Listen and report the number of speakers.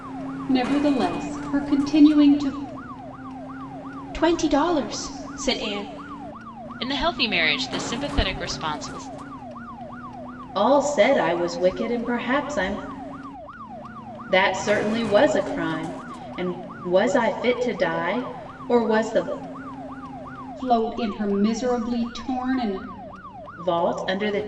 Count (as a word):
four